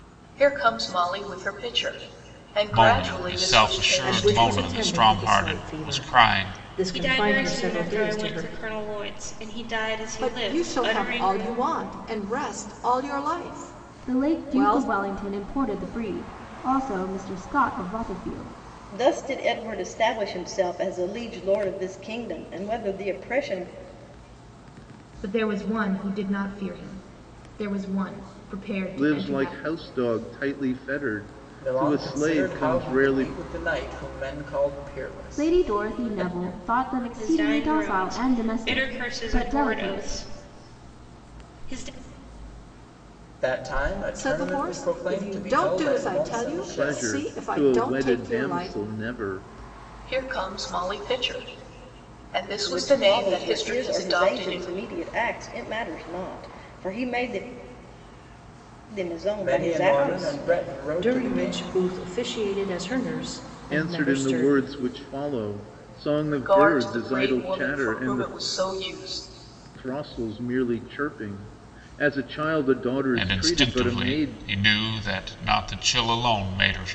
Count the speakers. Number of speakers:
10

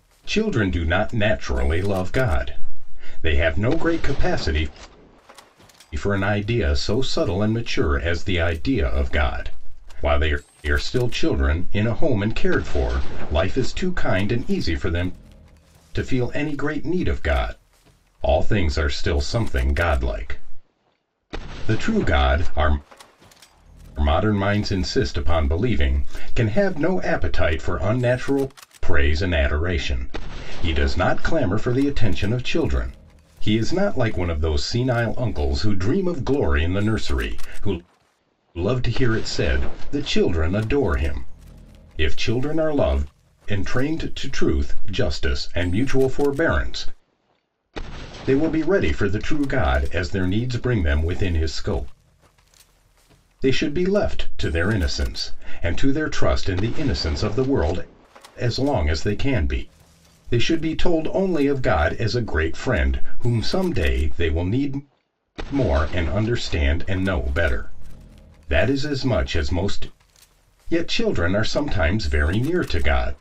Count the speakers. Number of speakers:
1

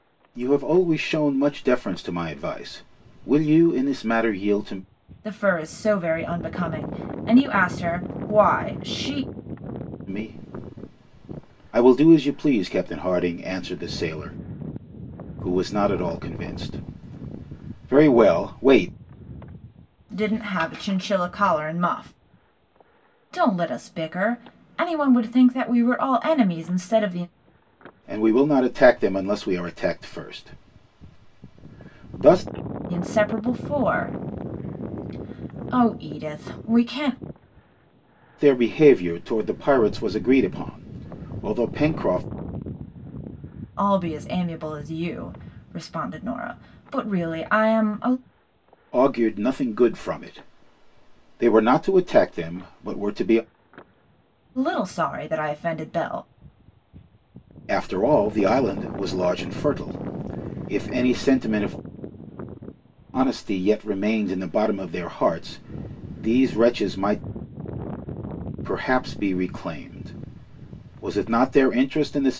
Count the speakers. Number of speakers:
2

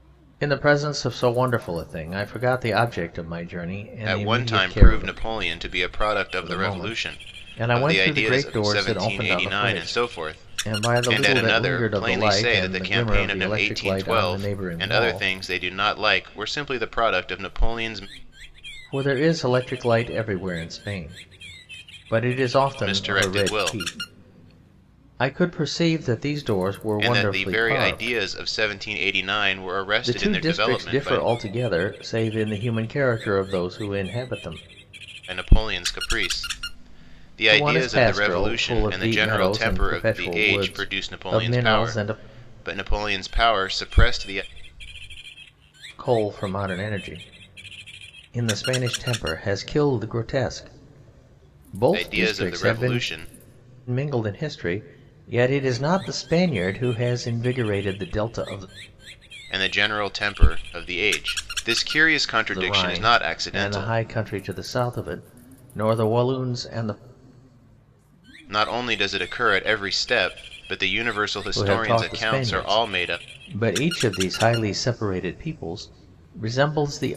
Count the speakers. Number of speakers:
2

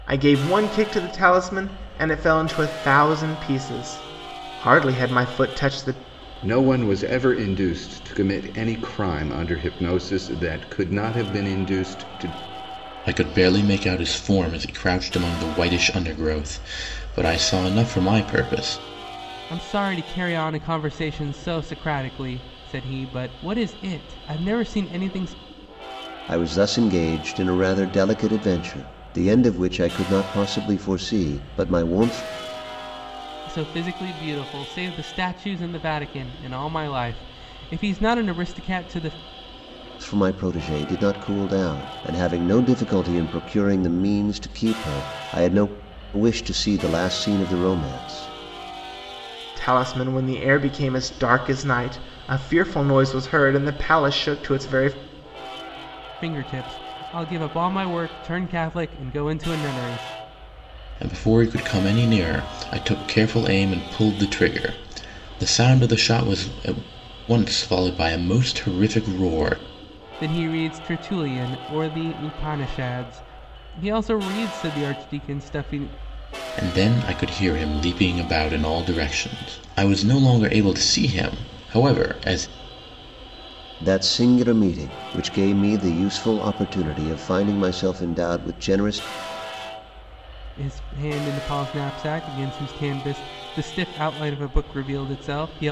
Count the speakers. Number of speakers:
5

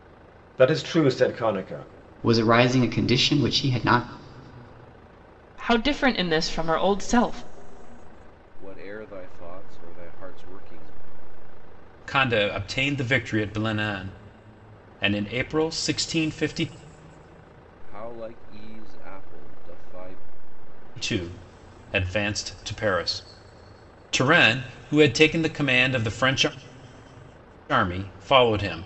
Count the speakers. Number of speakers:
5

